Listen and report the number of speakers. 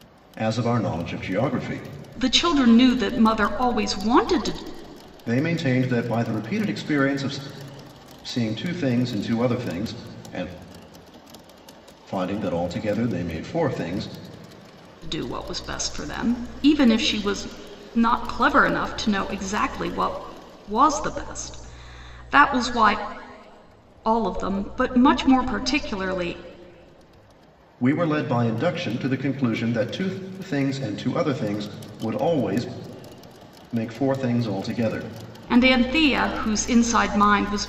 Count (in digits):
2